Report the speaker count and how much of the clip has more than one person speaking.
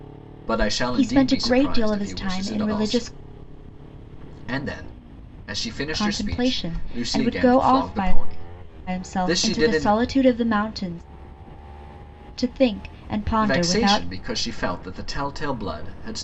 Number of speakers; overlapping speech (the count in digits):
2, about 39%